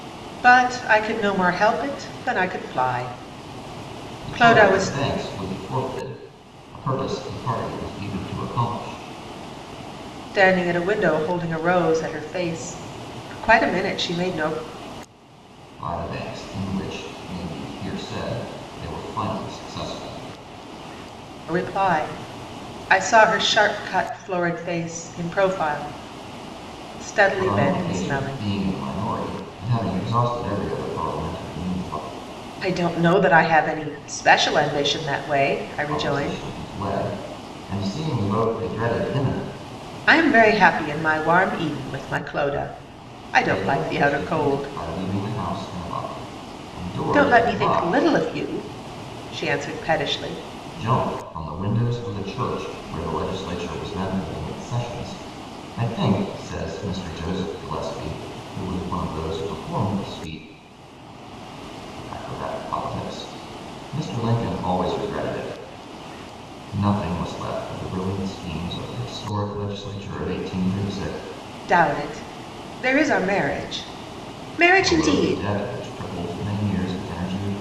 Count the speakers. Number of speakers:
2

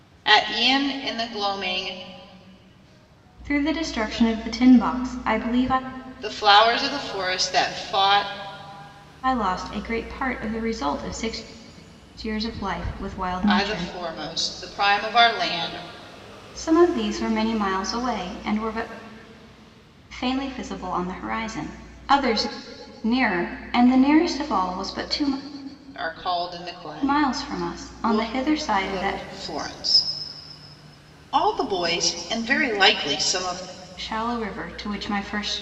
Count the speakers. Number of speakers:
2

